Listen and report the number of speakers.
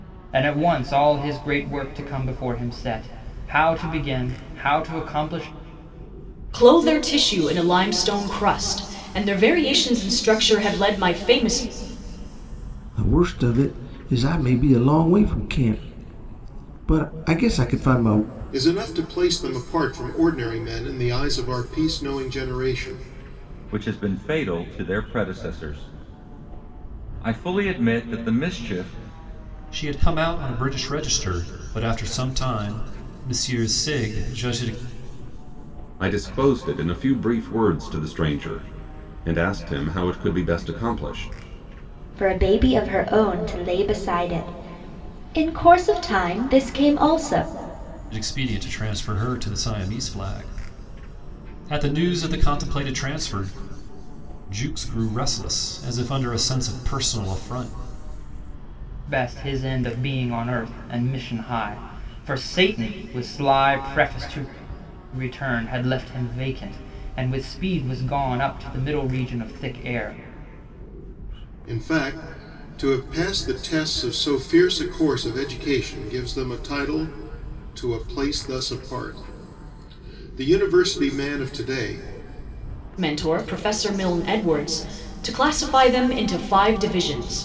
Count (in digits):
8